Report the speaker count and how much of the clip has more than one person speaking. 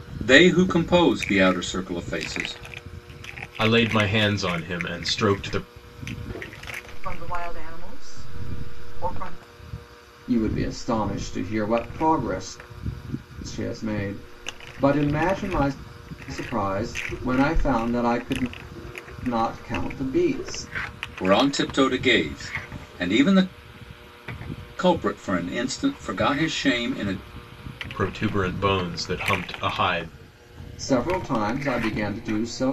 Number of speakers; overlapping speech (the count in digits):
4, no overlap